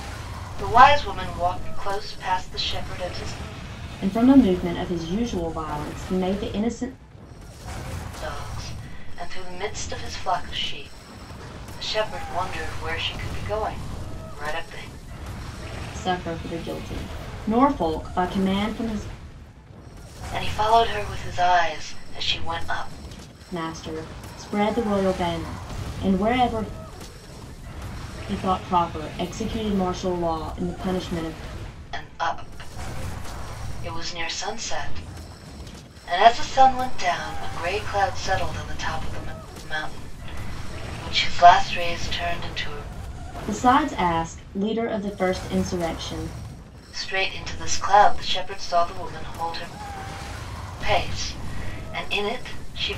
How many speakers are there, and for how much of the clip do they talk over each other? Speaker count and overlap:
2, no overlap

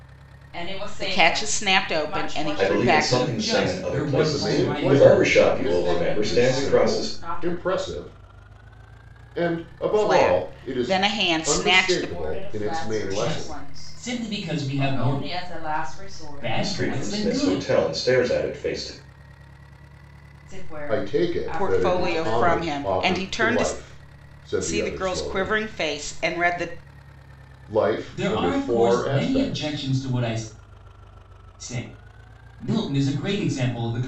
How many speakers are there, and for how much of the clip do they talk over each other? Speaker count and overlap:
5, about 52%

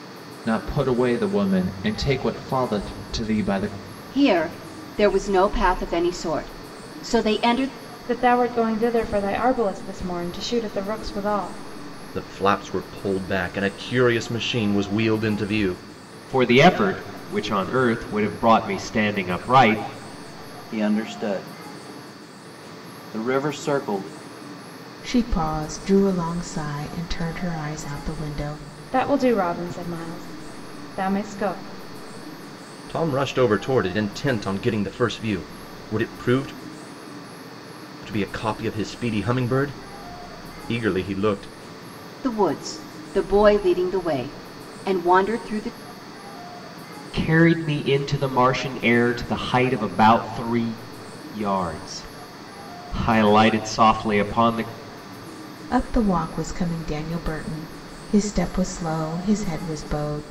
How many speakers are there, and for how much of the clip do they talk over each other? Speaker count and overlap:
7, no overlap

